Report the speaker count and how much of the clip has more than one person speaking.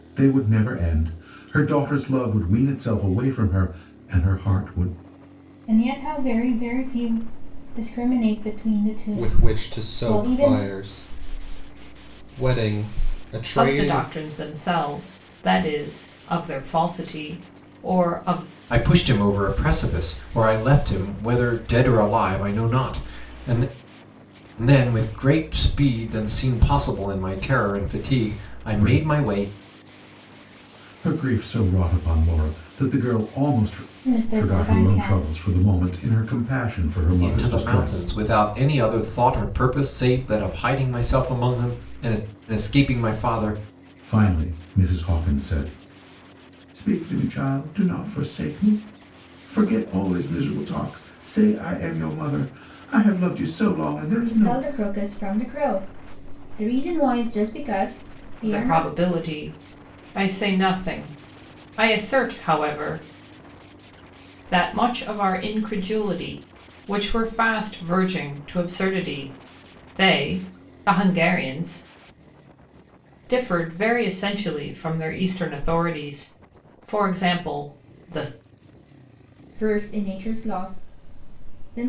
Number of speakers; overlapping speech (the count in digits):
5, about 7%